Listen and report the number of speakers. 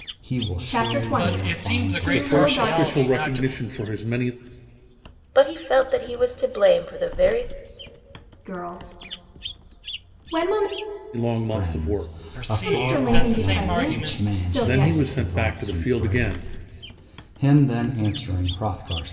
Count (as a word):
five